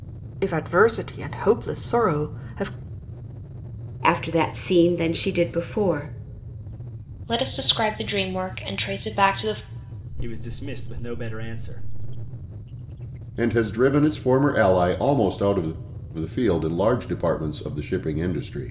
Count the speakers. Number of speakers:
5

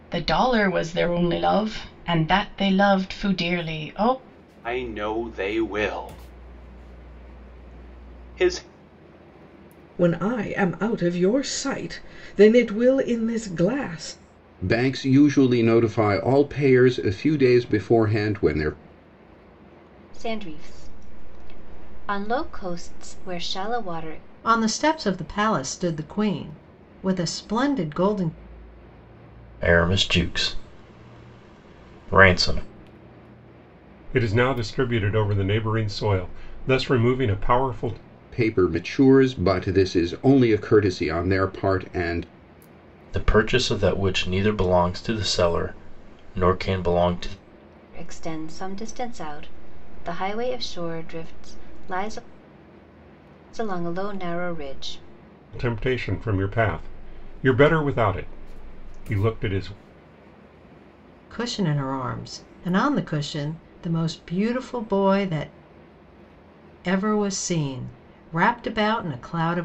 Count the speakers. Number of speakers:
8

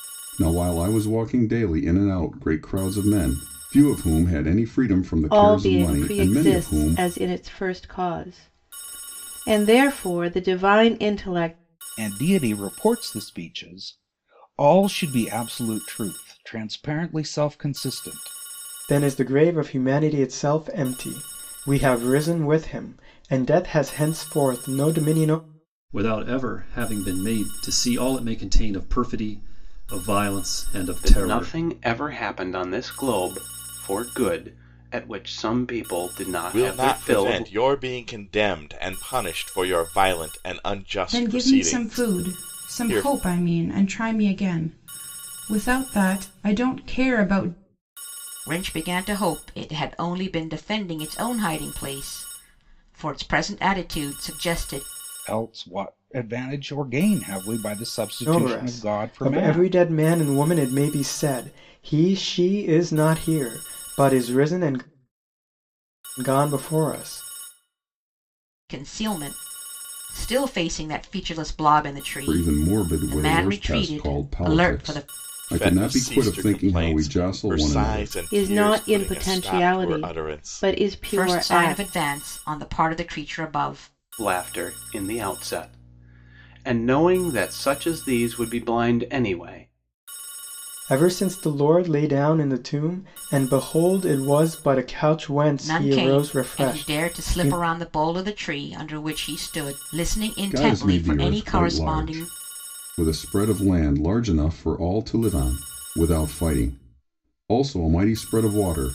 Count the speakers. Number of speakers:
9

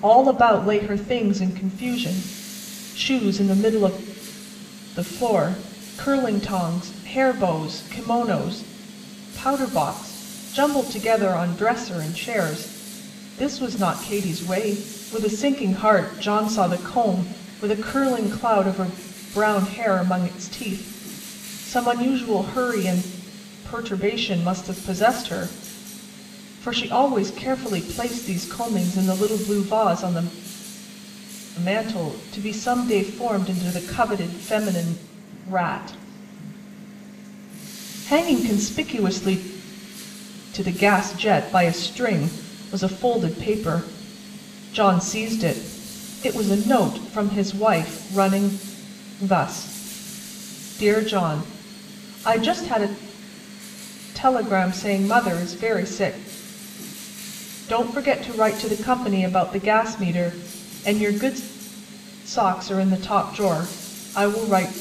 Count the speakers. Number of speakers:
1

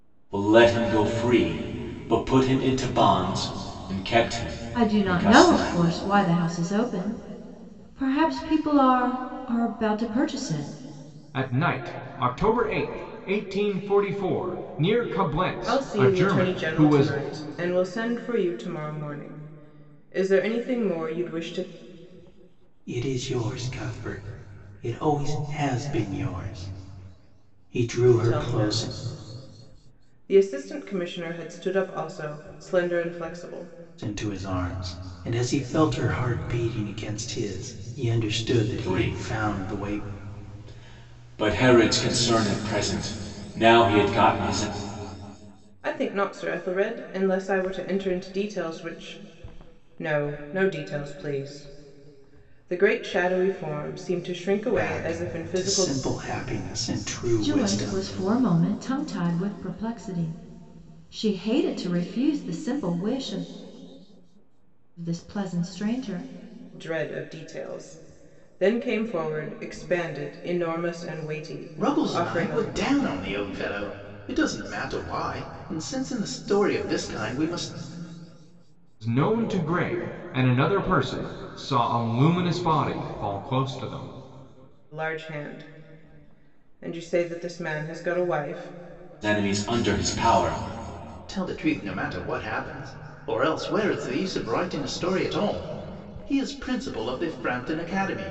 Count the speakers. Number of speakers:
5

